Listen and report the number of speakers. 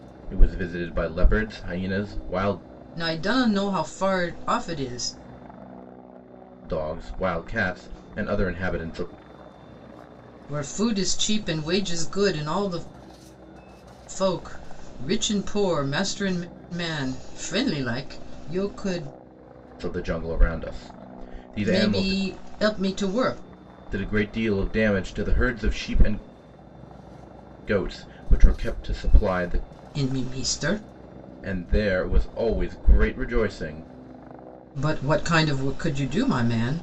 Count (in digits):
2